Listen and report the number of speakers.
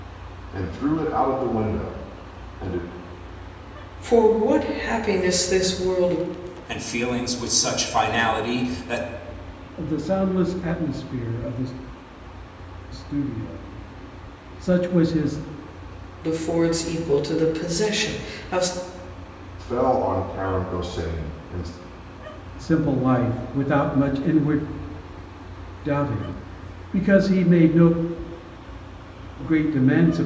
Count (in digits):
4